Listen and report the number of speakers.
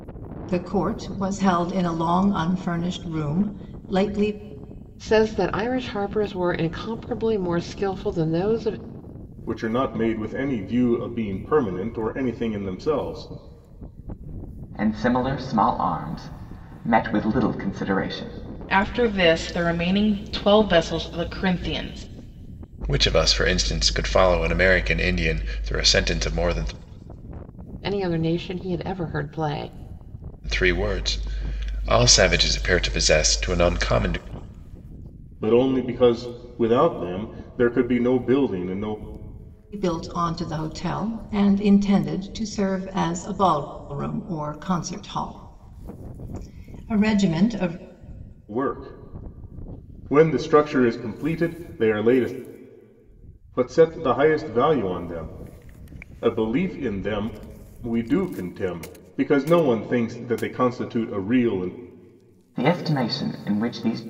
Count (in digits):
6